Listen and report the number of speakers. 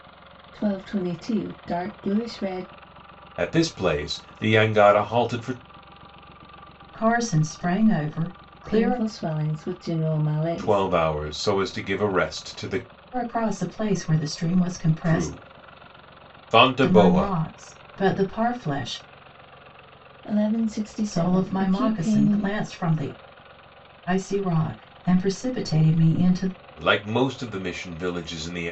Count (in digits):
3